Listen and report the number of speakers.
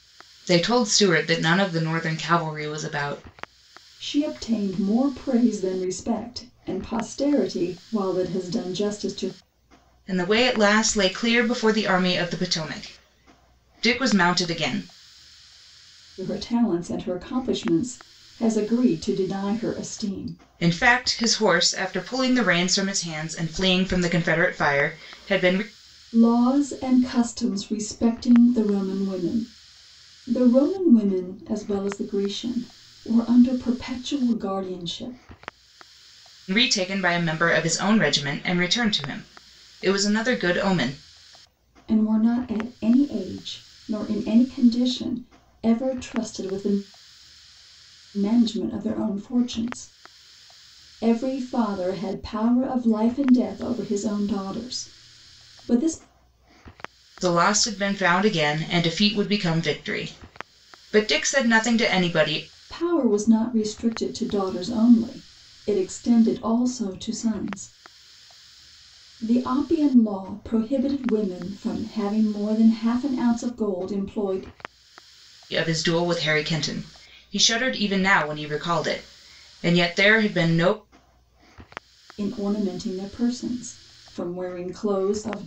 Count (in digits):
2